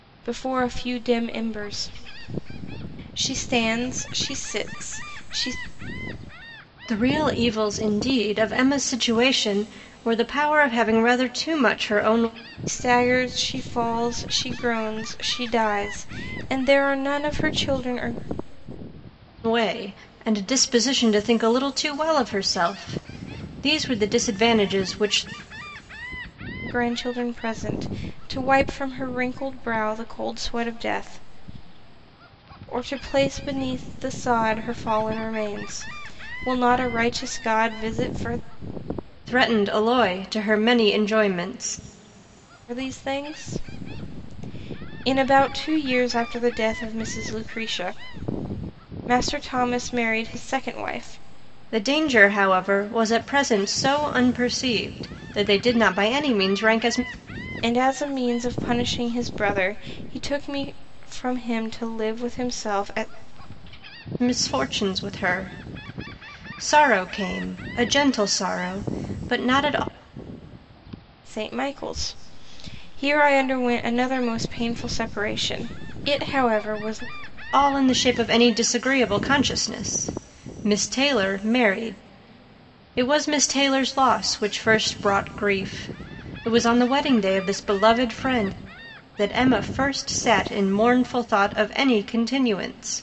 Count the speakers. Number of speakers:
two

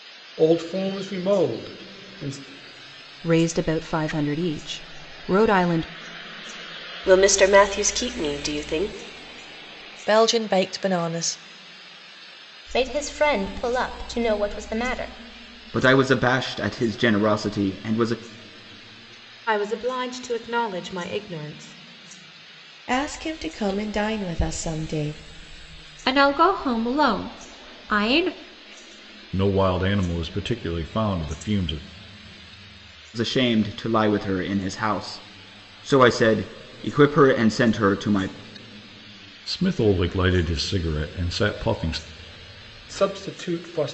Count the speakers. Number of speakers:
ten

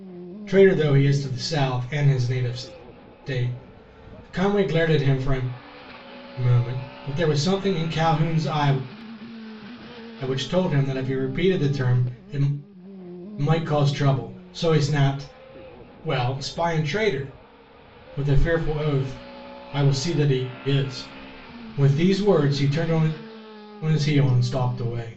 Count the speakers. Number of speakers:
one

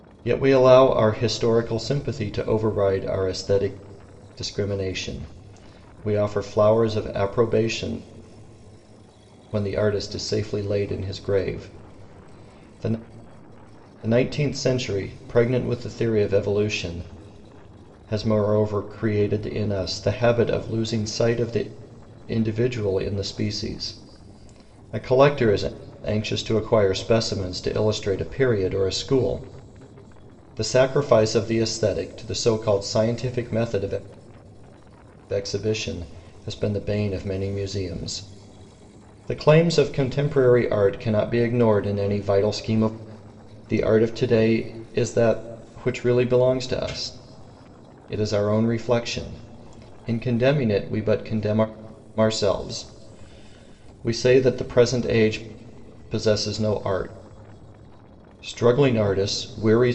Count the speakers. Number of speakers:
one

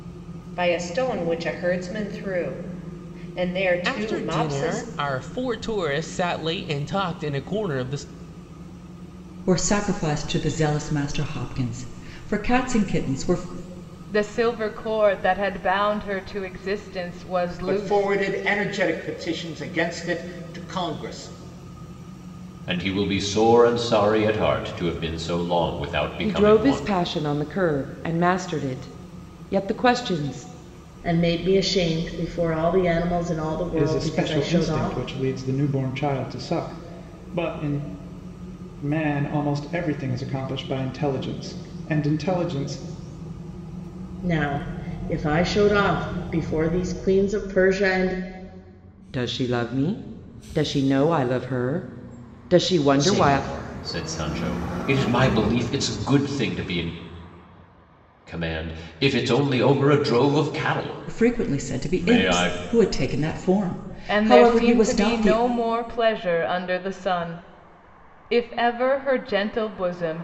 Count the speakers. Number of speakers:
nine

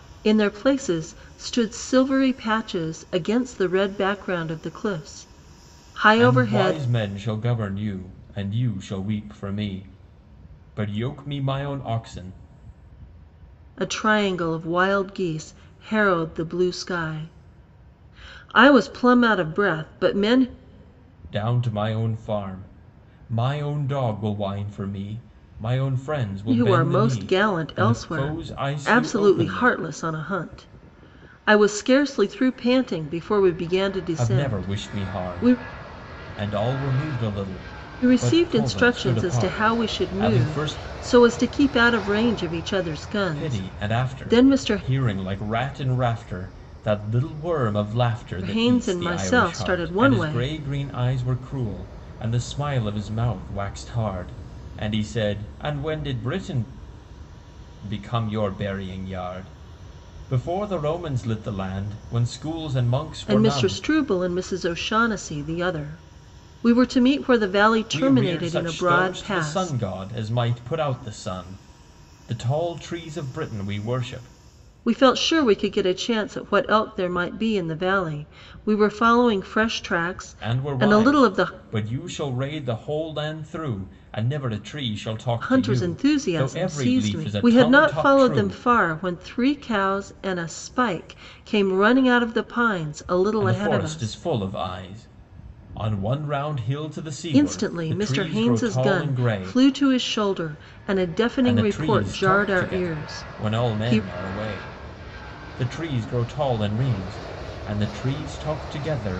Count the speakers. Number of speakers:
two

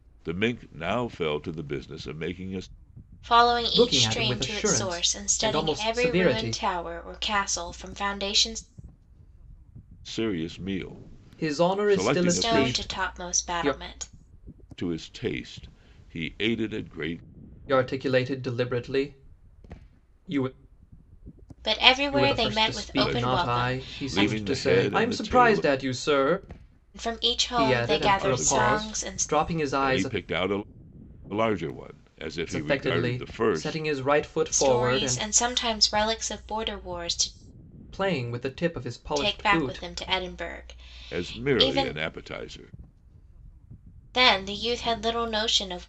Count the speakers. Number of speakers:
three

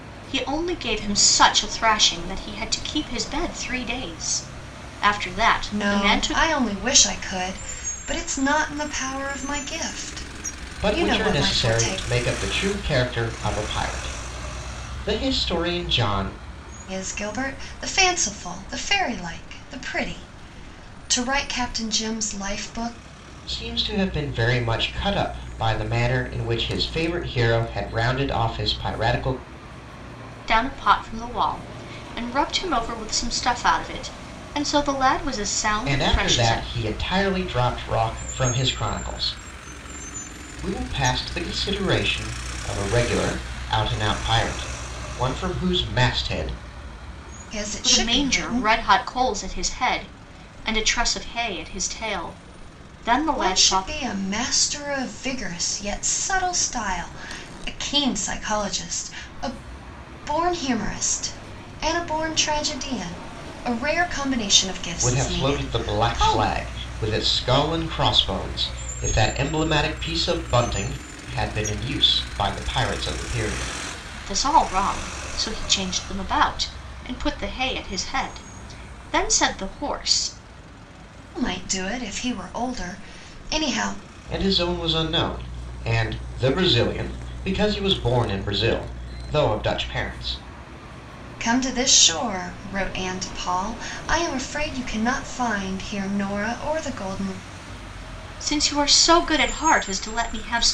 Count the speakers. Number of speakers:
three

